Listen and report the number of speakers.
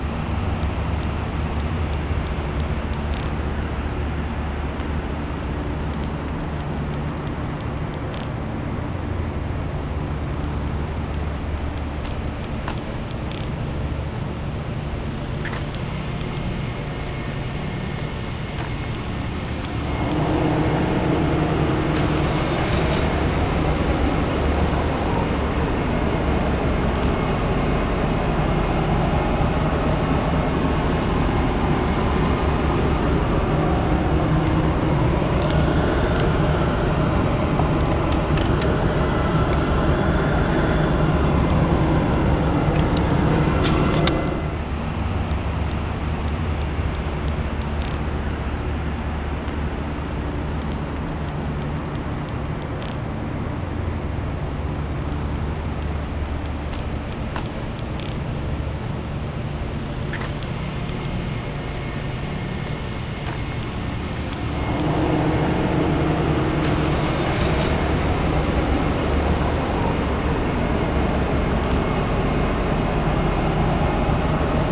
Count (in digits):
0